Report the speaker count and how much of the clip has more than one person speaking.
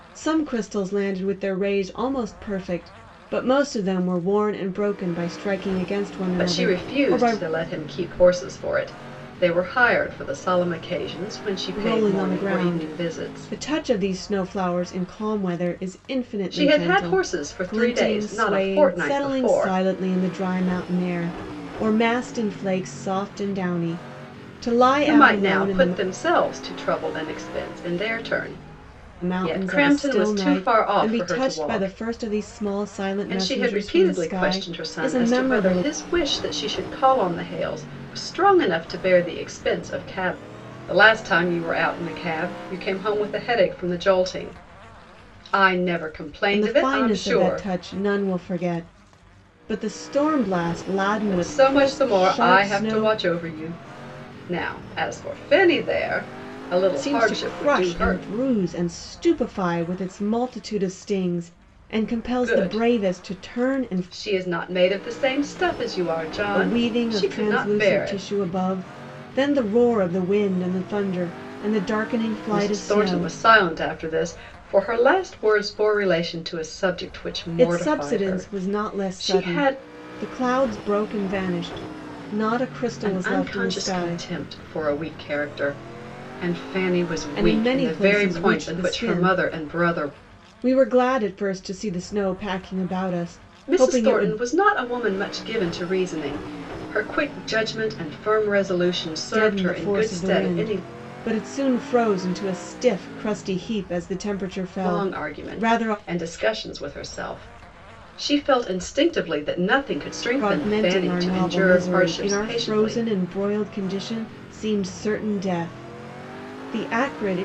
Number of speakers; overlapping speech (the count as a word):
two, about 29%